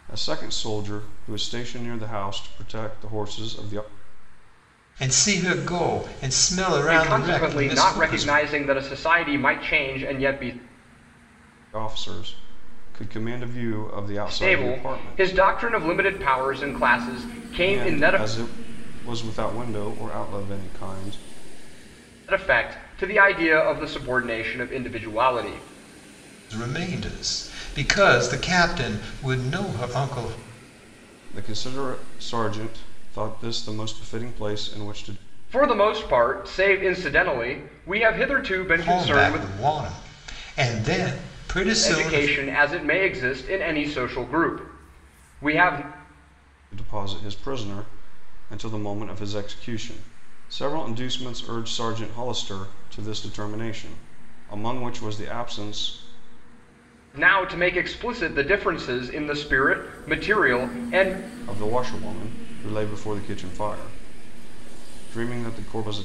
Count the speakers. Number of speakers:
three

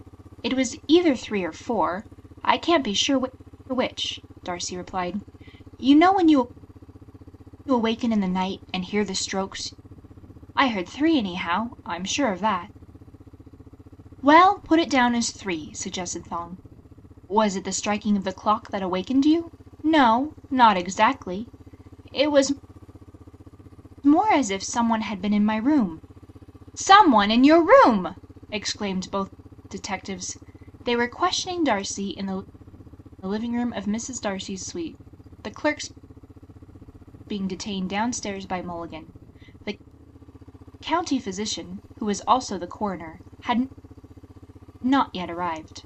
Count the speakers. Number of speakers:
one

